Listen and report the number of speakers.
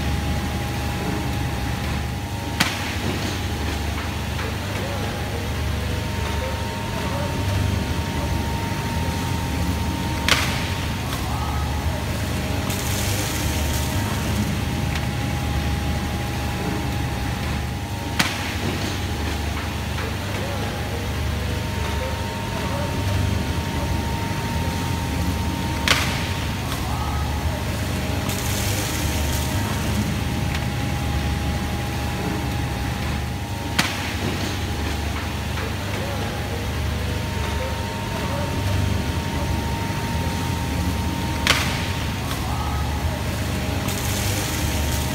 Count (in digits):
0